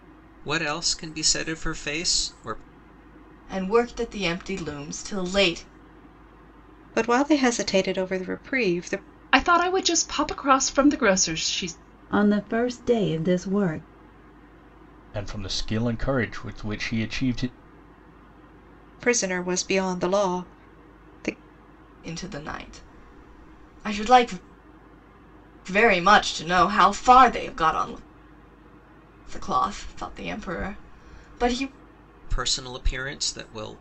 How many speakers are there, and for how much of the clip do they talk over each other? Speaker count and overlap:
6, no overlap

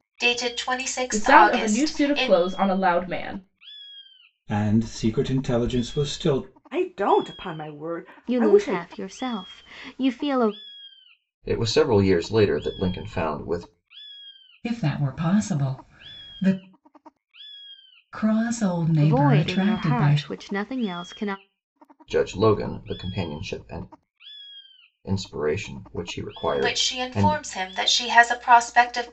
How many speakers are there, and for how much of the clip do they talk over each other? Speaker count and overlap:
7, about 14%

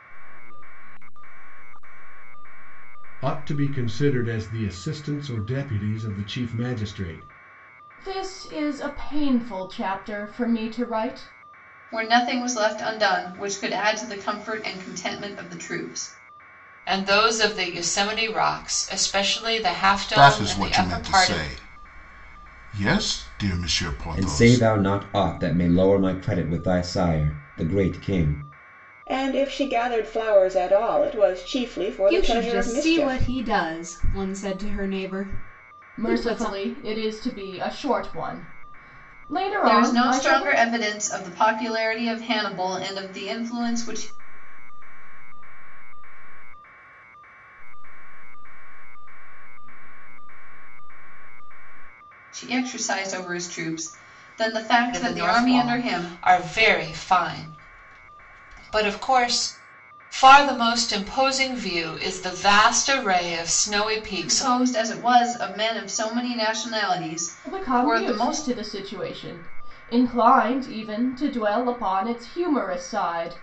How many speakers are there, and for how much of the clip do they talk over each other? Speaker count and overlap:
9, about 12%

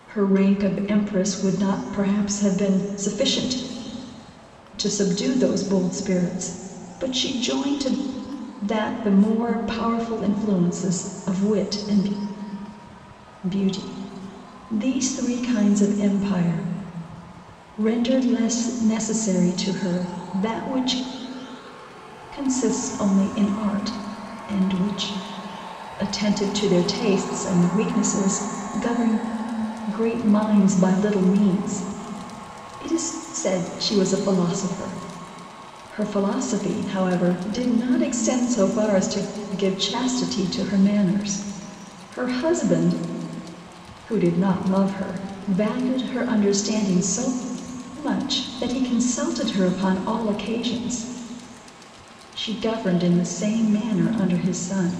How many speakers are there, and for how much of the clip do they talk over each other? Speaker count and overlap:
1, no overlap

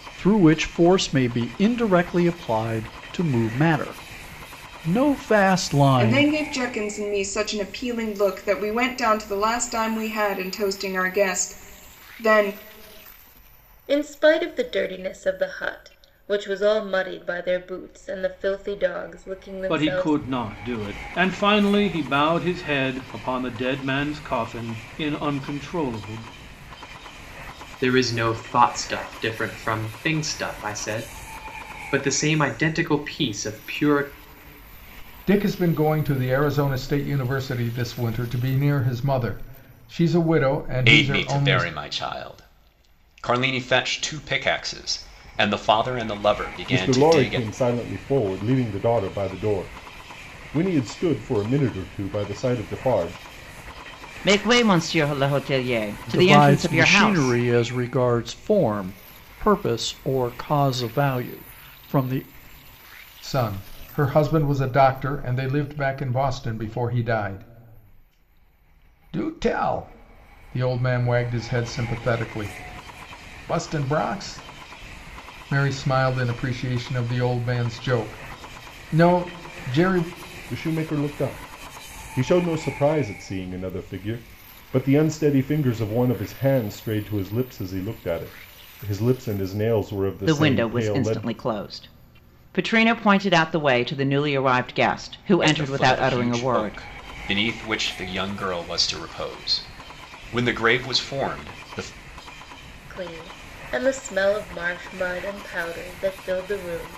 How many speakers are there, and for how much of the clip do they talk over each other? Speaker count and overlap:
9, about 6%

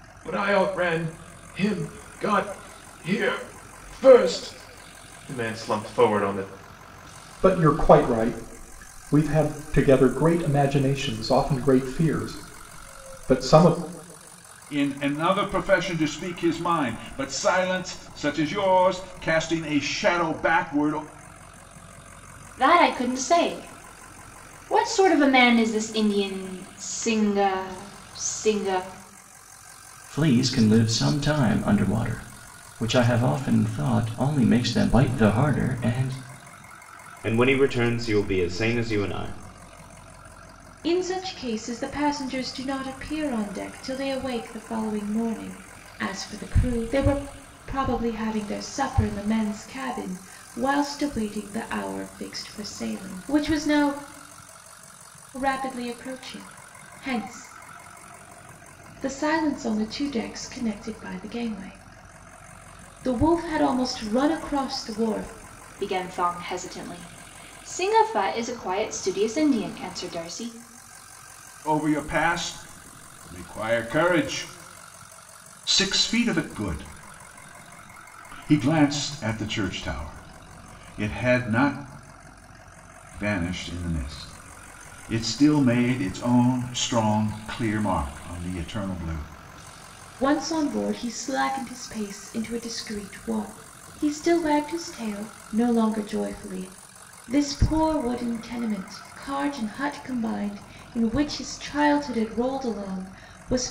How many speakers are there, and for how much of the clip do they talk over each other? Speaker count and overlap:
7, no overlap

